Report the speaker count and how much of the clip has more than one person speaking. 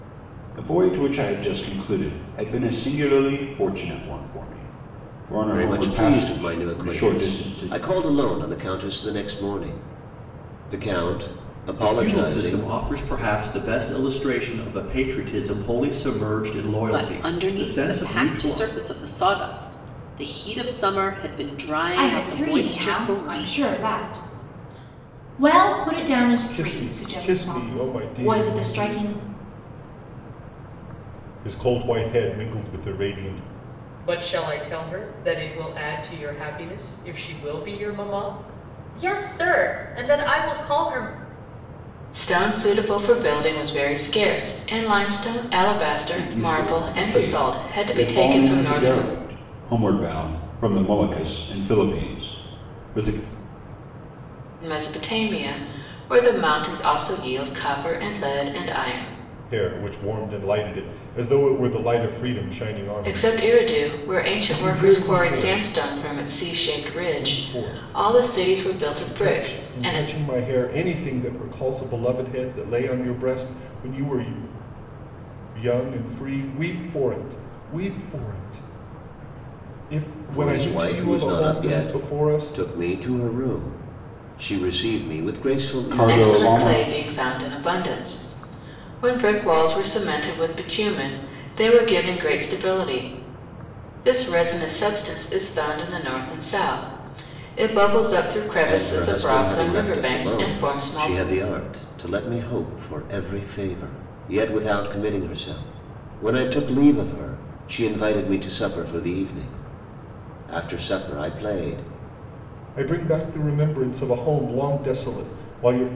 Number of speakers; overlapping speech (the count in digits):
8, about 21%